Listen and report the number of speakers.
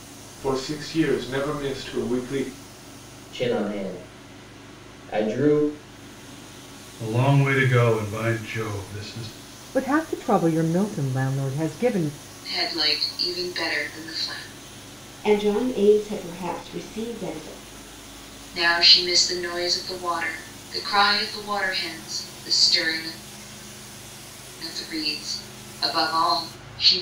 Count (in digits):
6